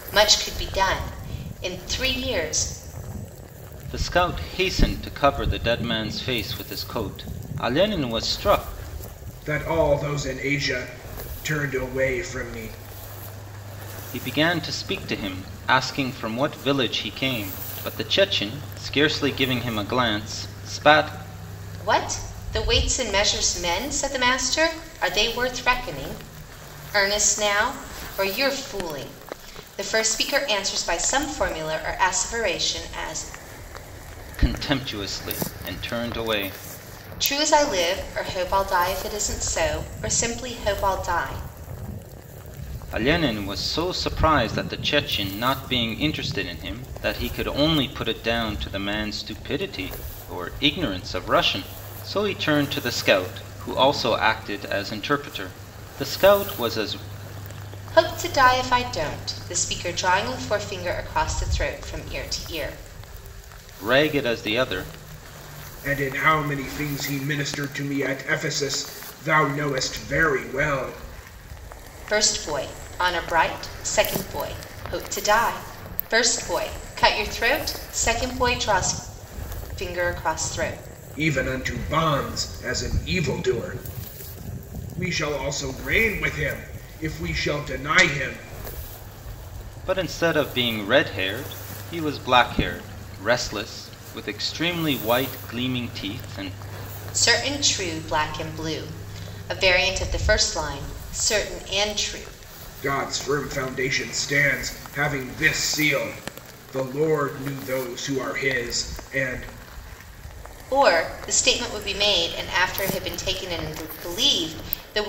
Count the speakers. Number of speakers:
three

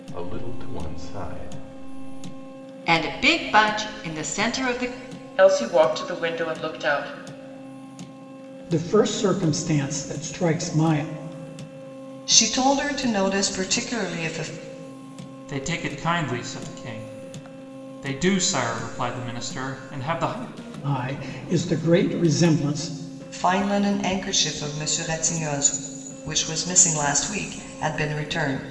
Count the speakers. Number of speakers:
six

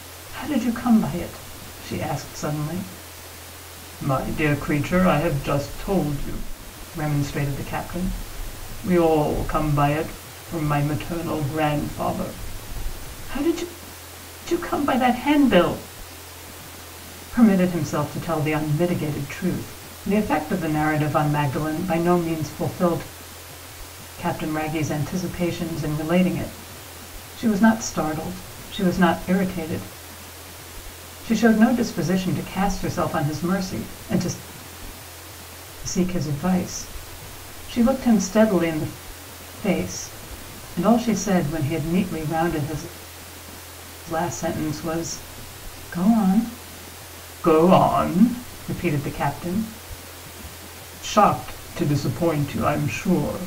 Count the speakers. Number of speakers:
one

